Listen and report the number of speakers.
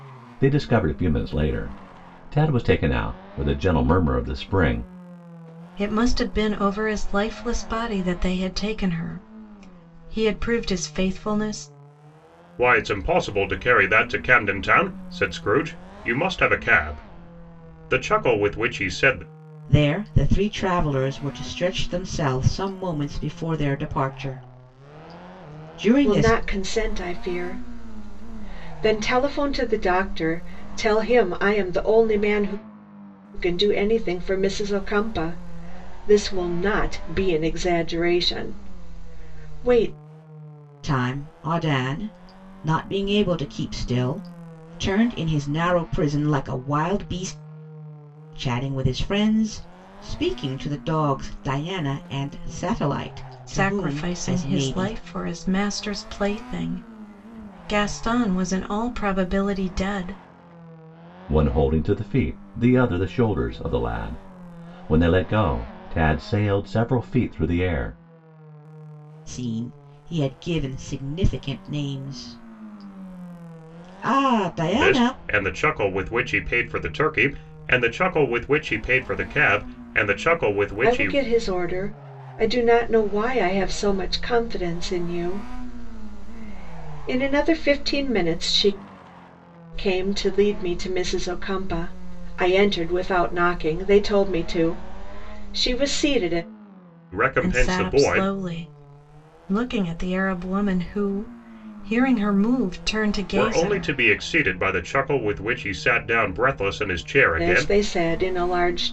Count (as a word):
five